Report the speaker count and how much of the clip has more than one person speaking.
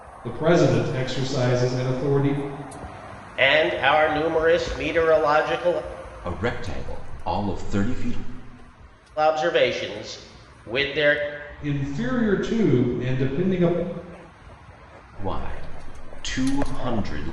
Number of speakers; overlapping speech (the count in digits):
3, no overlap